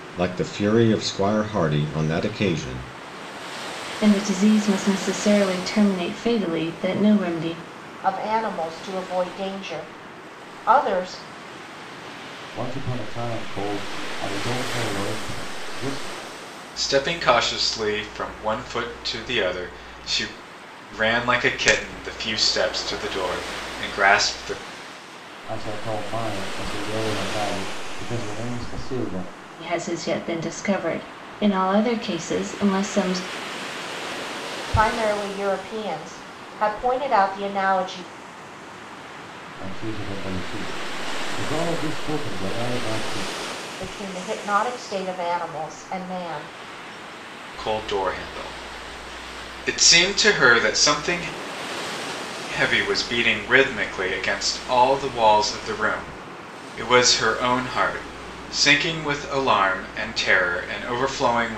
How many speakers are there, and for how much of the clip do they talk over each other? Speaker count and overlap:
five, no overlap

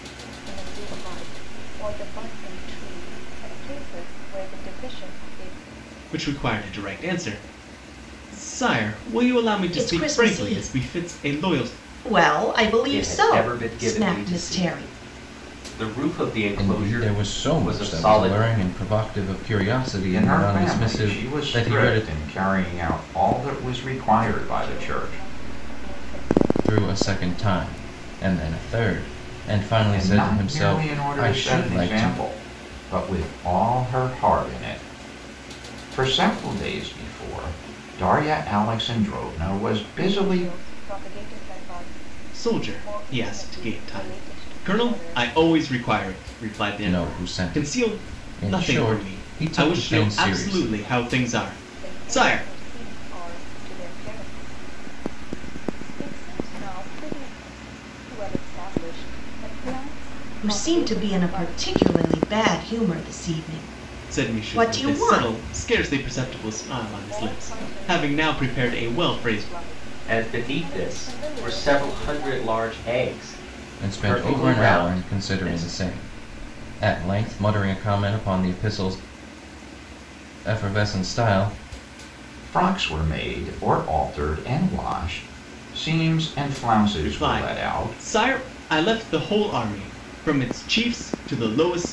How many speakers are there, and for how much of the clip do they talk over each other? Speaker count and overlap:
six, about 33%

